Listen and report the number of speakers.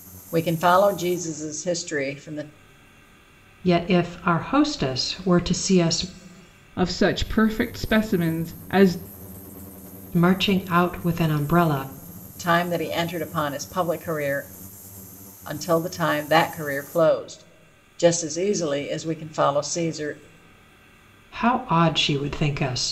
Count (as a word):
three